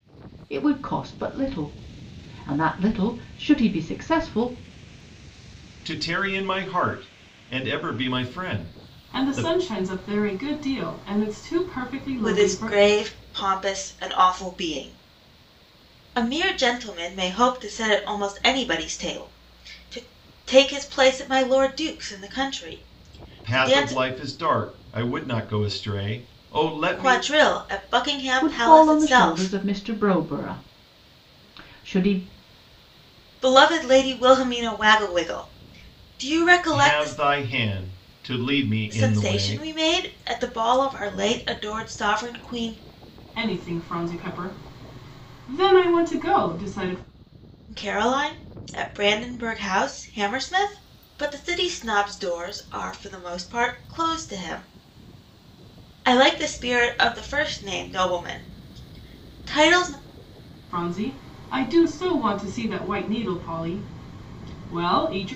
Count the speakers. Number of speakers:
4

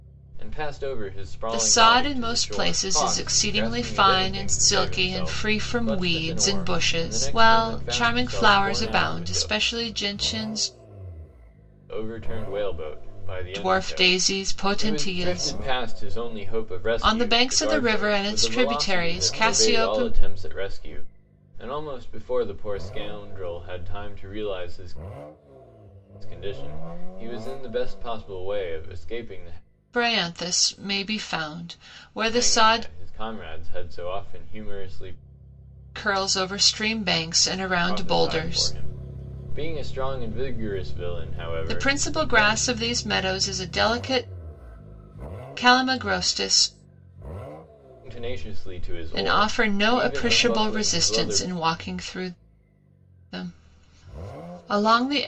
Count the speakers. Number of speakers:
2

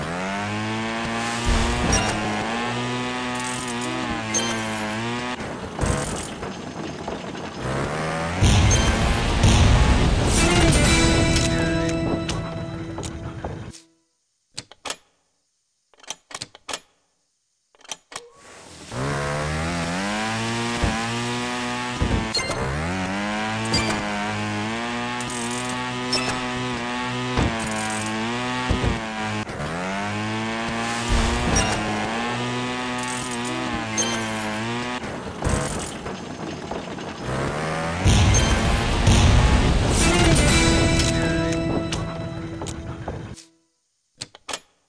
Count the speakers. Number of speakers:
0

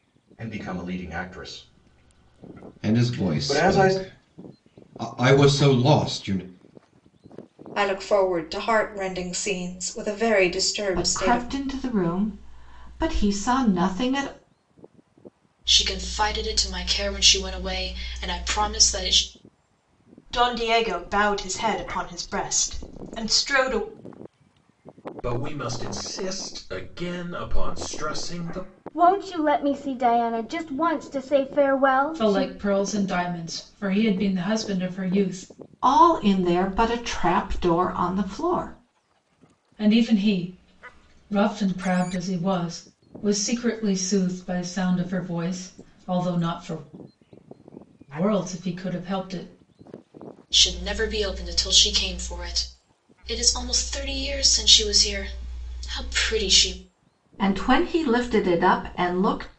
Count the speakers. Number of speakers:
9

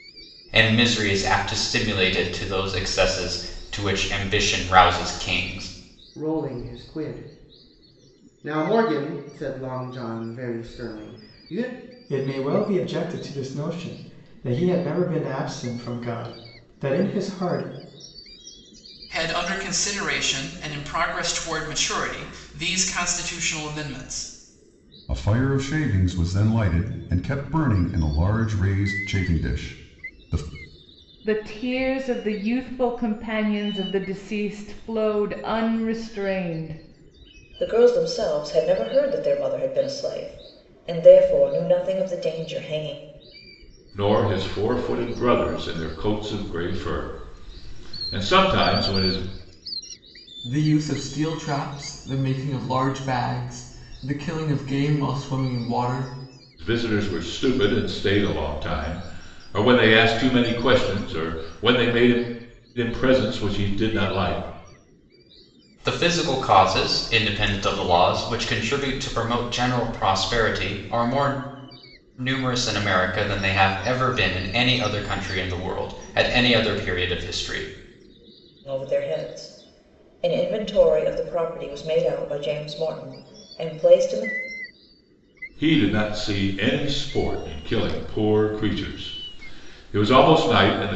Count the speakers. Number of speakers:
9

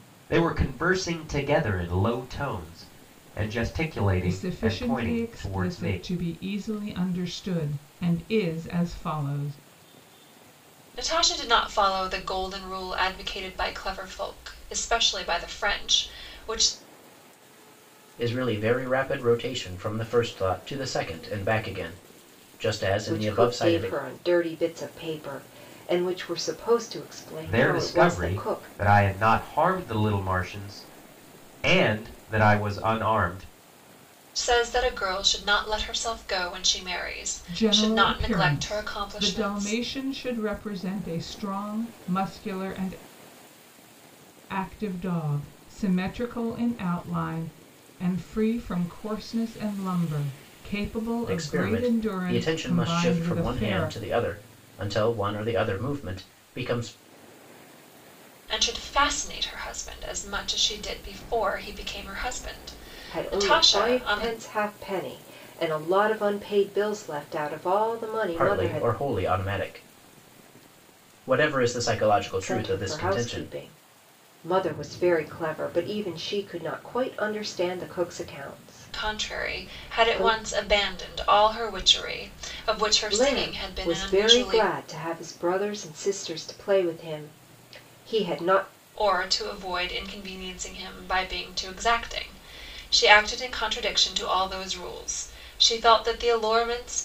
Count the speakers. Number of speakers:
5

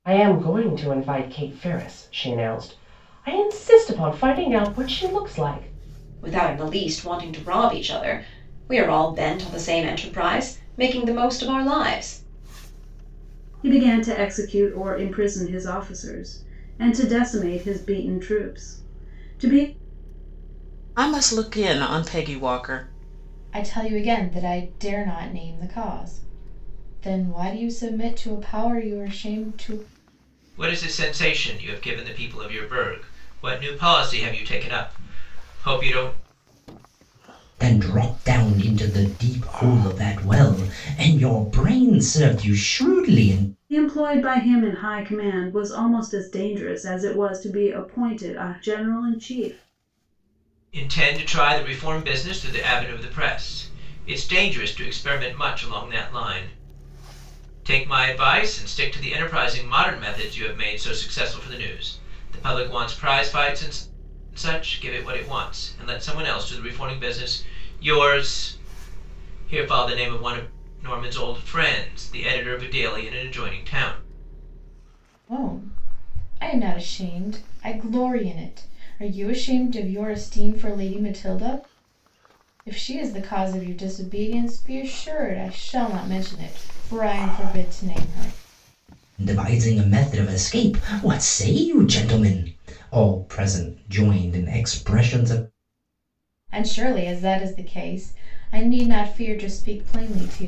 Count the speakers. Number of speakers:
7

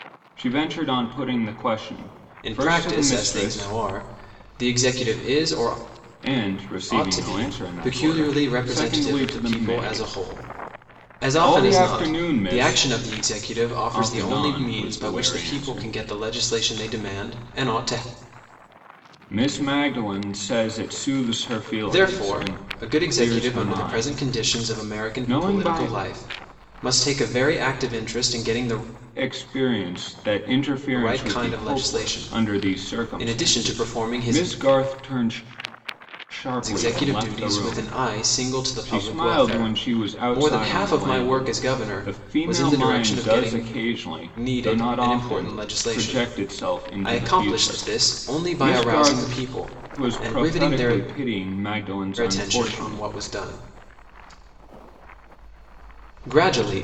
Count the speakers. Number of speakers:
2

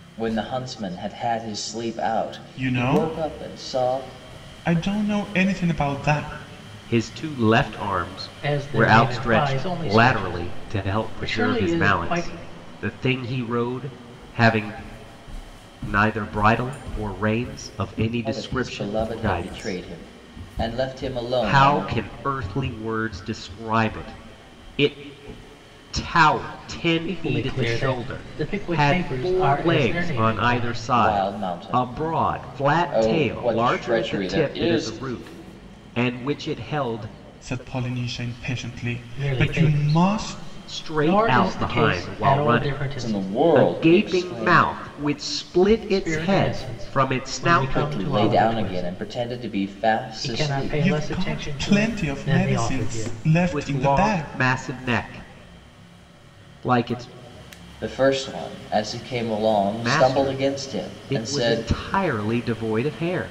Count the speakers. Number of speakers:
4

